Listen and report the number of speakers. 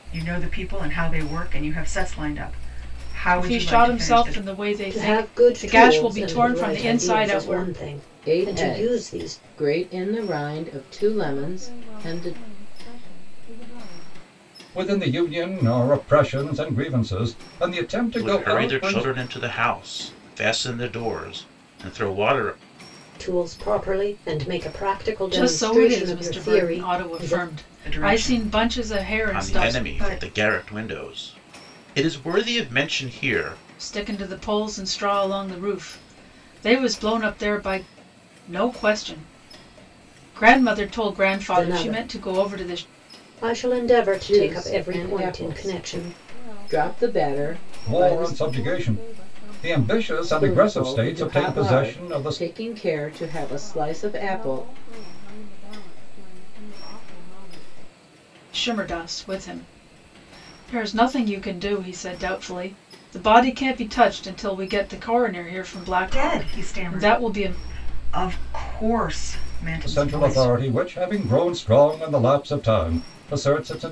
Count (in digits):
7